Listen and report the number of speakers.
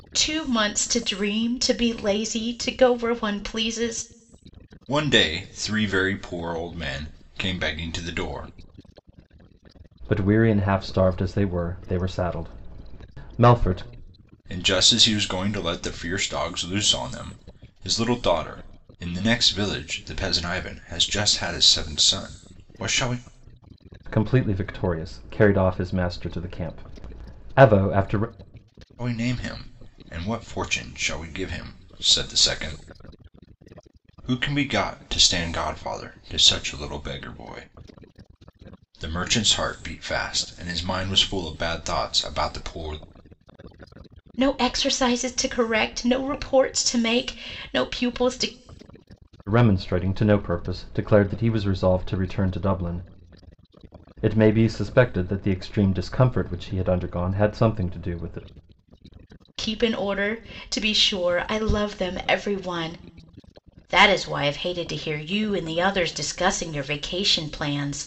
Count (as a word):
three